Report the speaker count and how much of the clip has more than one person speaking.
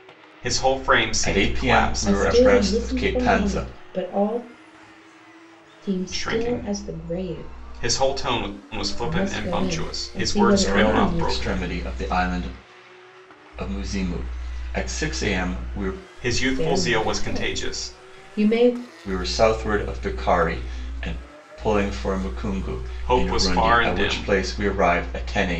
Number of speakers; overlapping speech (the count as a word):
three, about 37%